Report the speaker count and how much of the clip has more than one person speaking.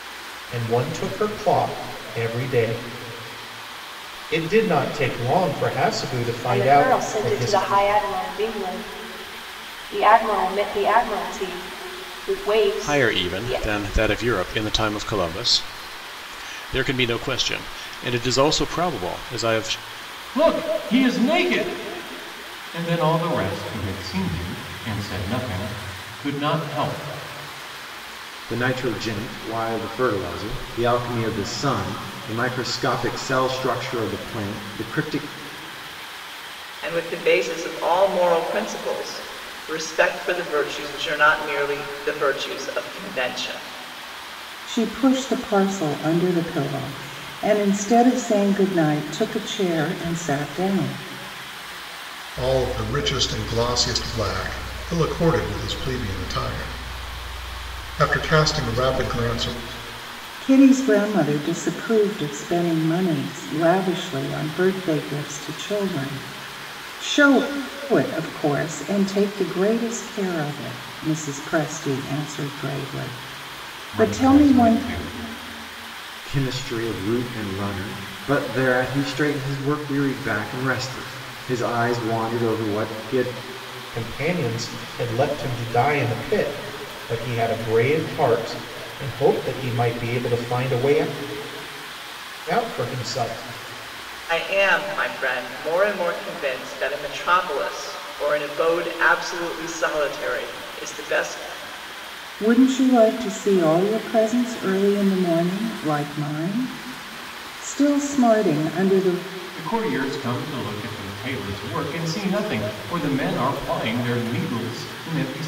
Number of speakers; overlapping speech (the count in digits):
8, about 3%